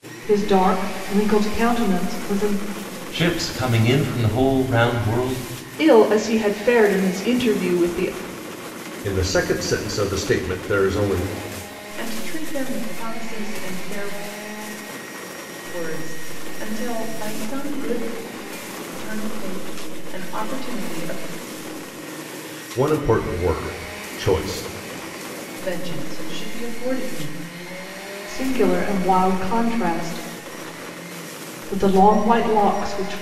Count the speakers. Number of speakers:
5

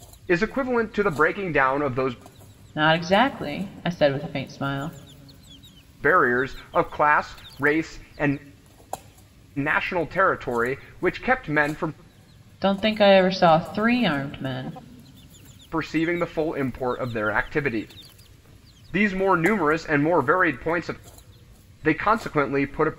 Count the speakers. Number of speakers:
2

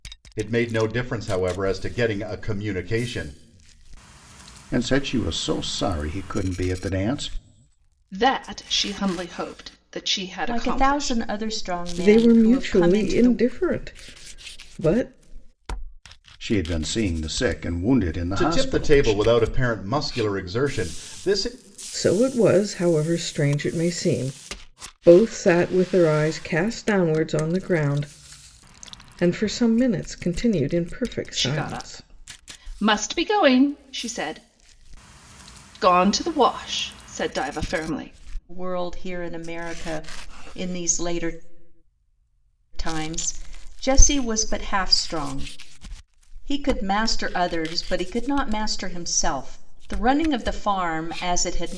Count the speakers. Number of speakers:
5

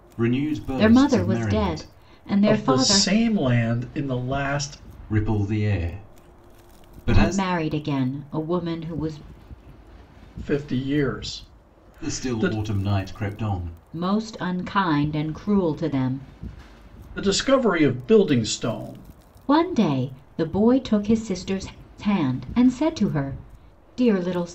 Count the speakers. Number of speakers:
3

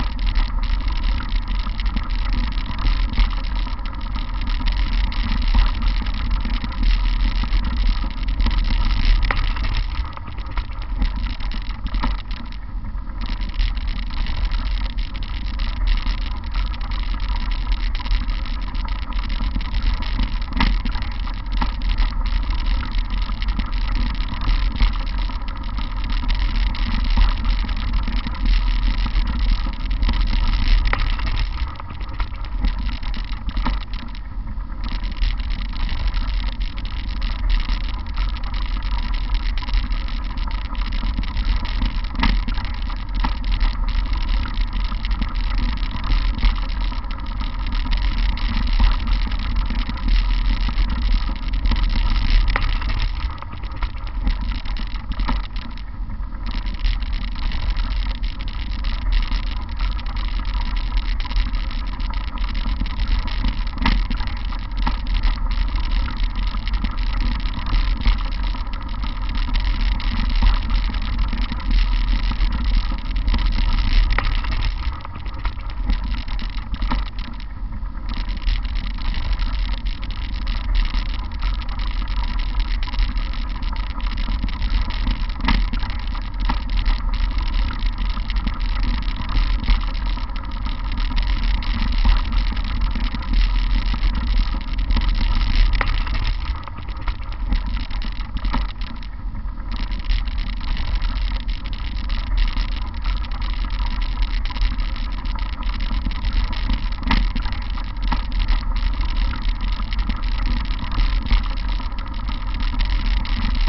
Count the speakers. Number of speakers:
0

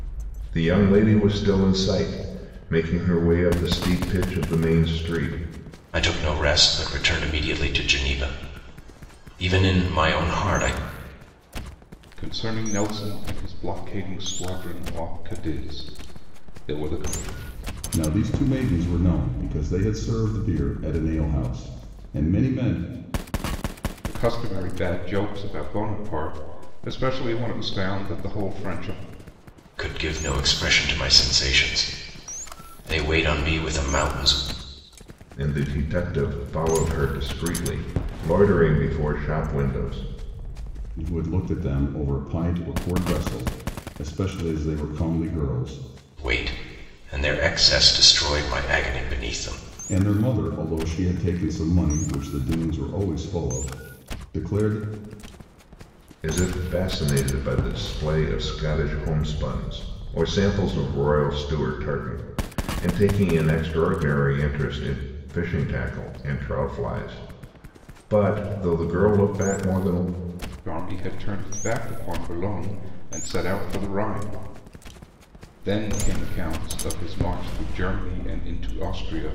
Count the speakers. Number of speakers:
4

